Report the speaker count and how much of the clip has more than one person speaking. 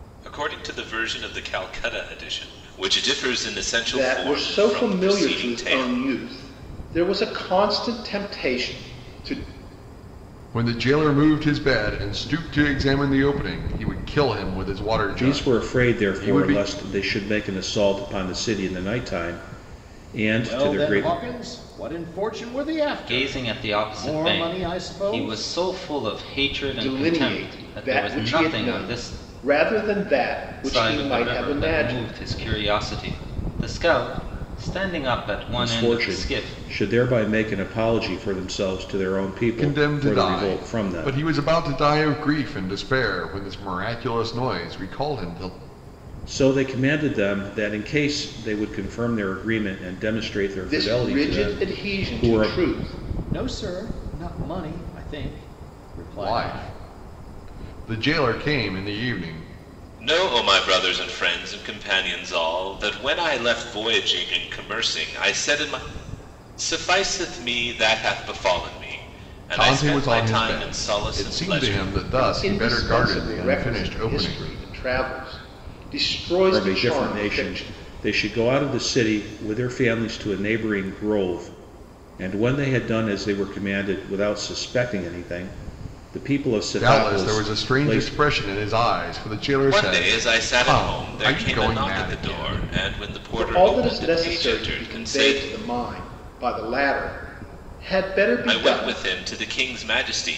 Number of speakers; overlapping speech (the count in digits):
6, about 29%